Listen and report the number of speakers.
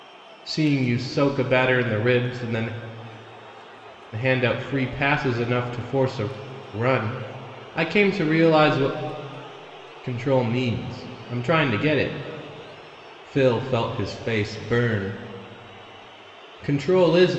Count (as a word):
one